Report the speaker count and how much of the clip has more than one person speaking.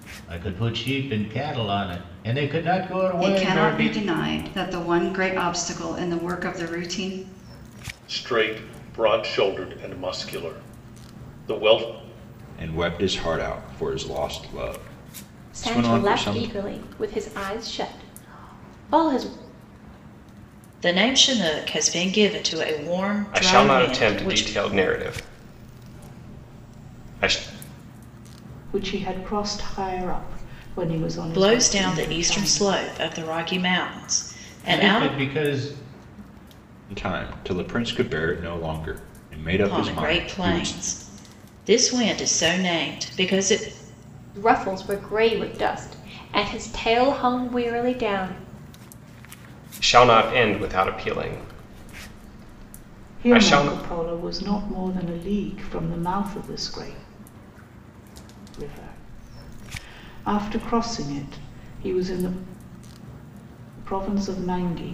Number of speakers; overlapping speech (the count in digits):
8, about 10%